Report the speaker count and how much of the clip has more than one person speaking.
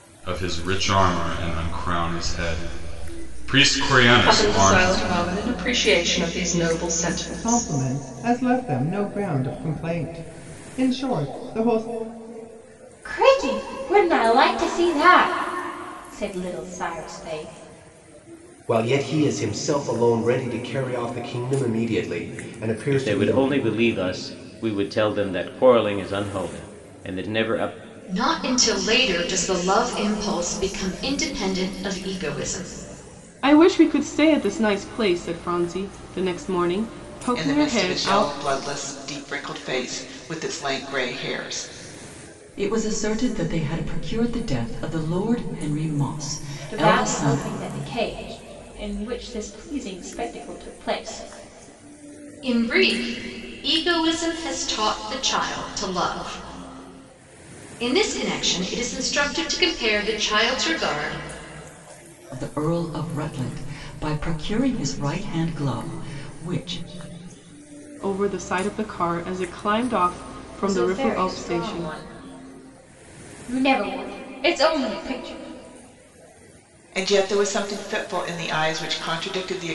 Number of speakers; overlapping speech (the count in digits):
10, about 6%